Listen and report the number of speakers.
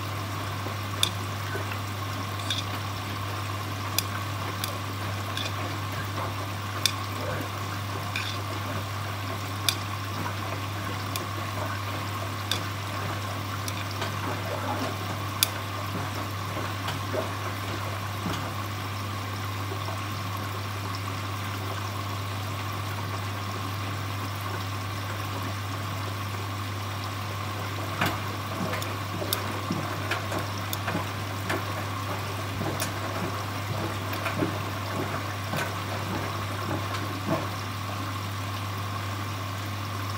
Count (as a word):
zero